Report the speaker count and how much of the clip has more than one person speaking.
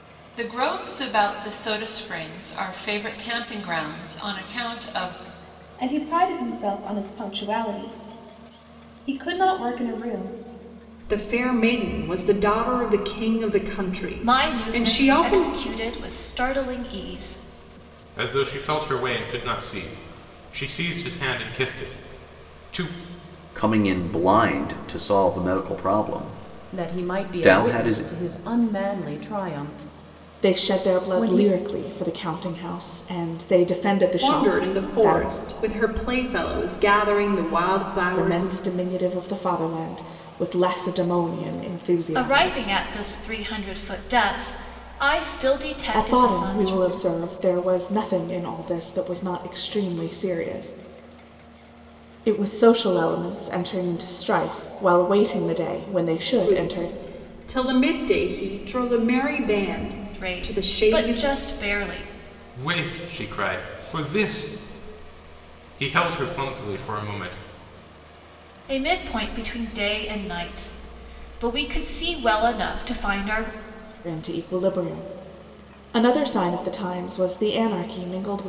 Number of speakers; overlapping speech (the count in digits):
8, about 11%